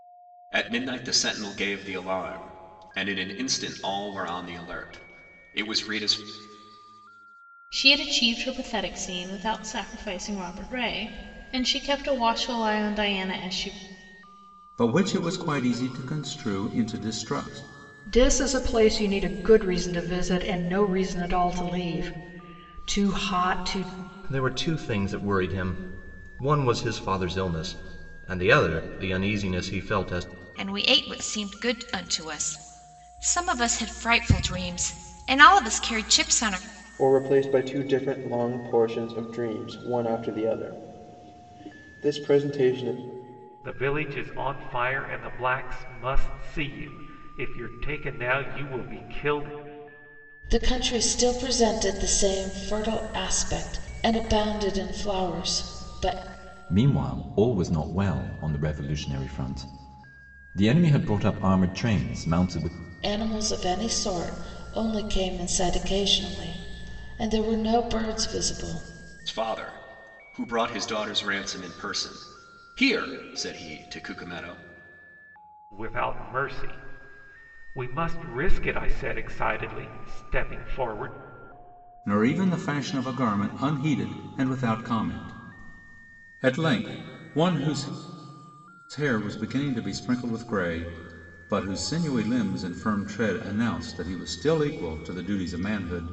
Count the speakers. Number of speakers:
10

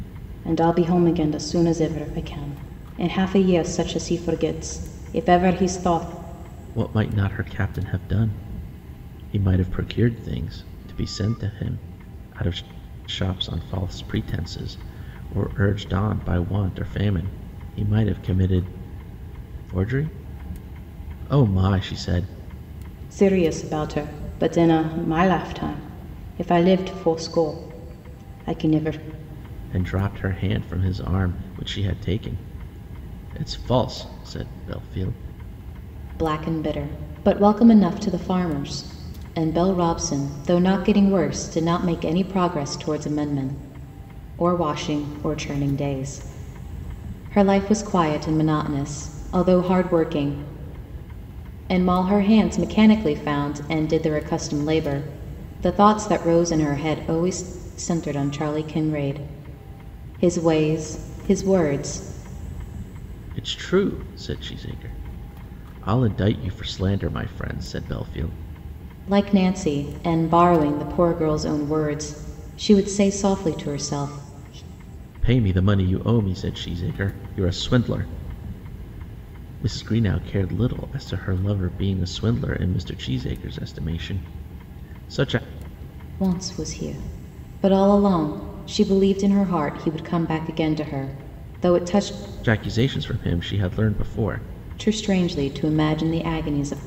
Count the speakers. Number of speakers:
2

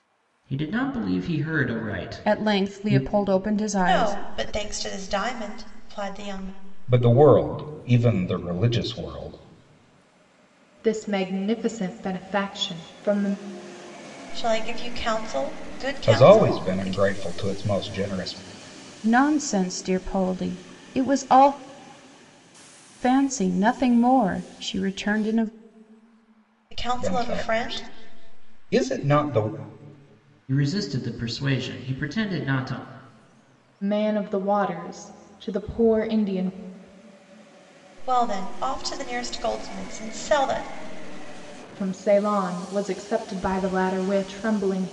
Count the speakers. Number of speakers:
5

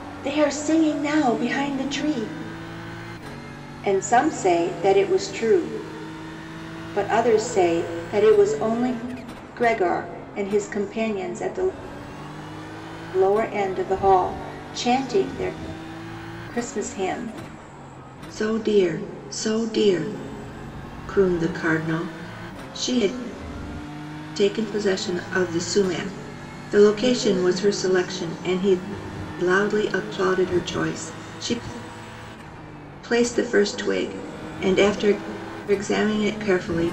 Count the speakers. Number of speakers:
1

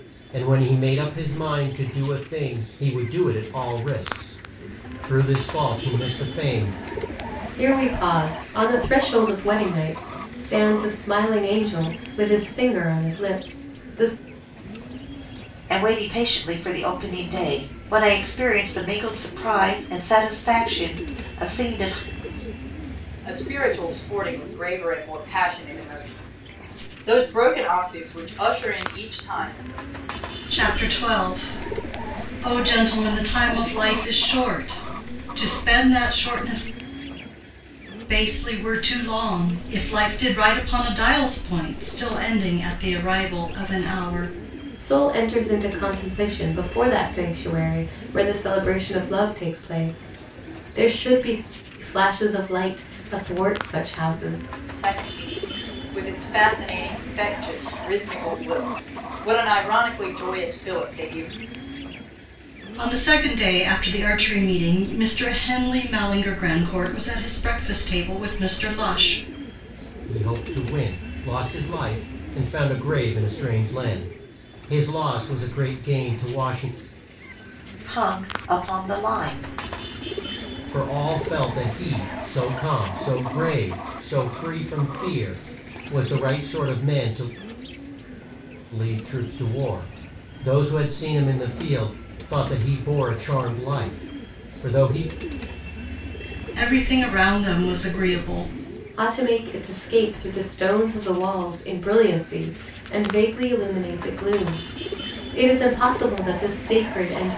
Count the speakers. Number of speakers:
5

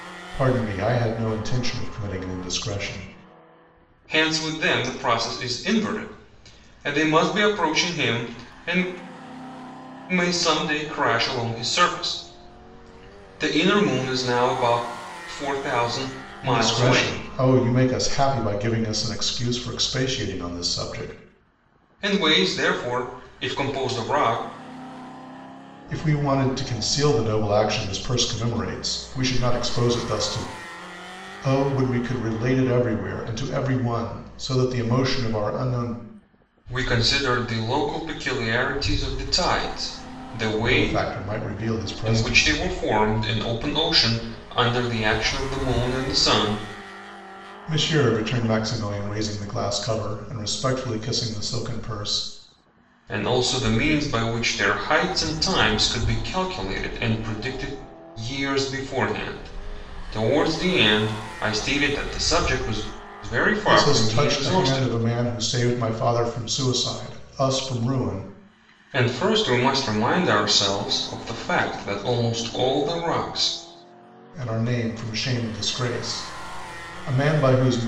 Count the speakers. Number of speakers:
2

